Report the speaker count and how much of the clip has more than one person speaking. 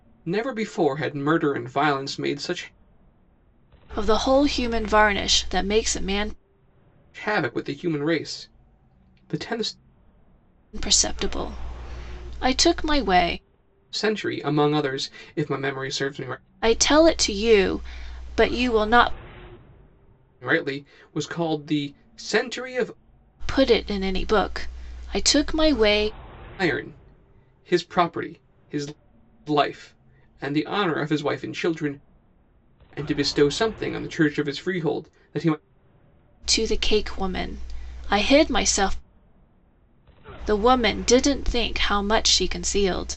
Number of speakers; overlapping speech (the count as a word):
two, no overlap